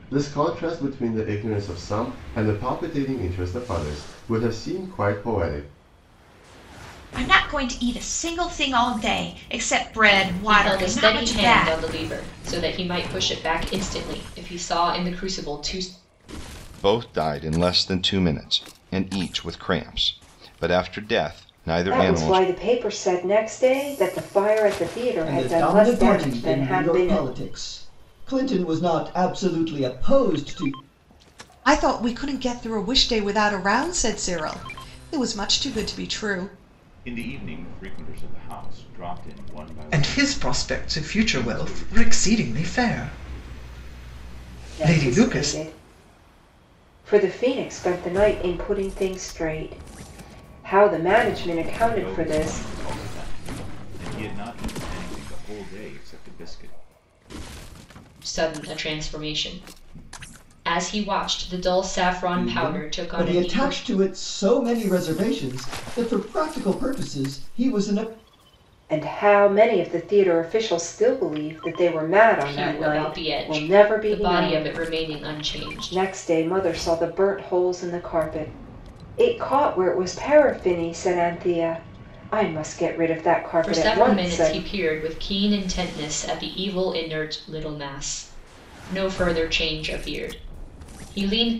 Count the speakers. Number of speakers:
nine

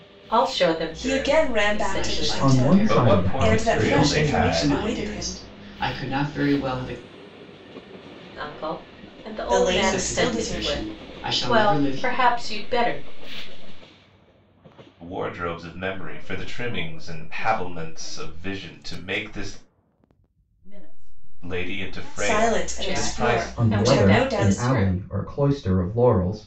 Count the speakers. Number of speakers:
six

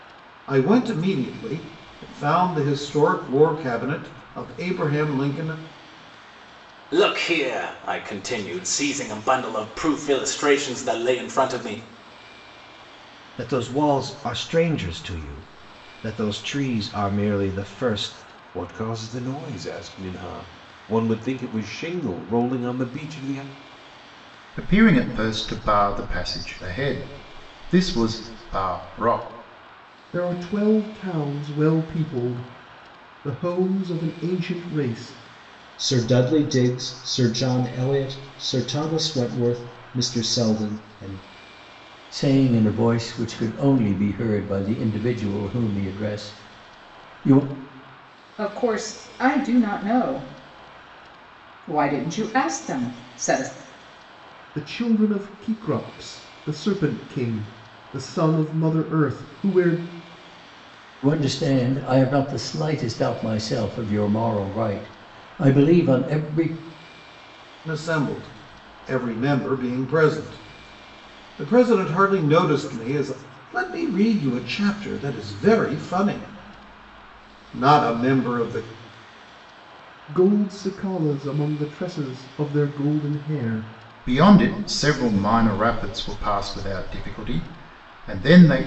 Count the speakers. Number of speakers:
nine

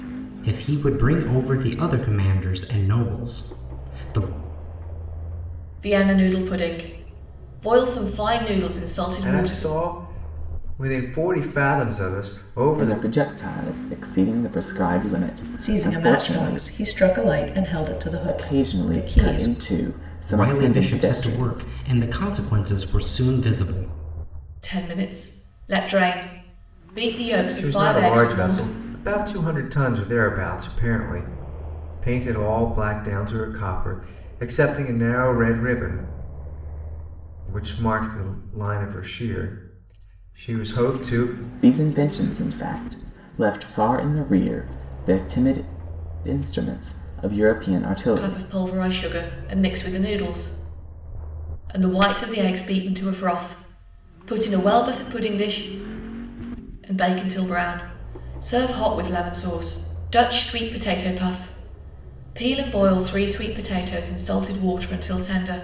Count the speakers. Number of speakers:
five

